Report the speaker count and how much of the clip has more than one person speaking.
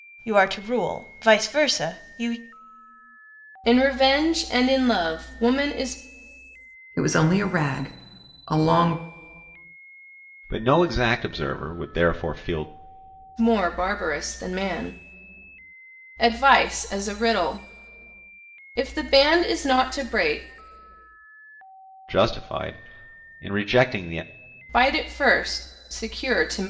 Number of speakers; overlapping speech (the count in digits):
4, no overlap